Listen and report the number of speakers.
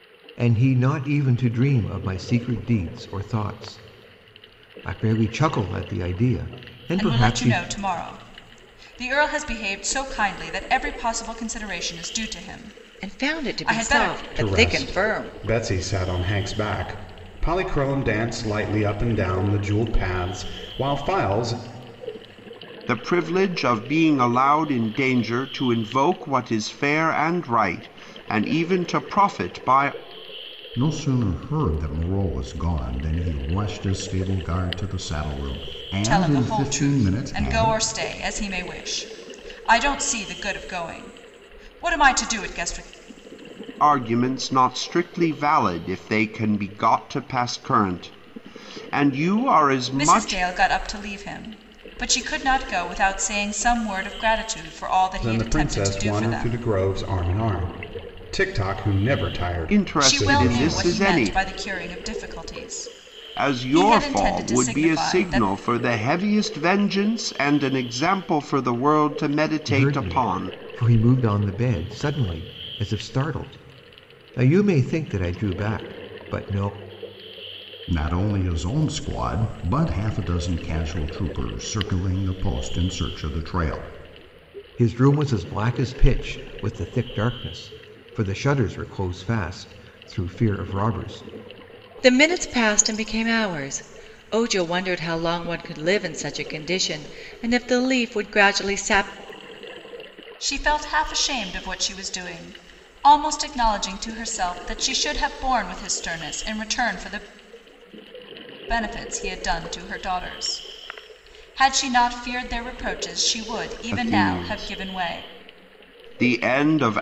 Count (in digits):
6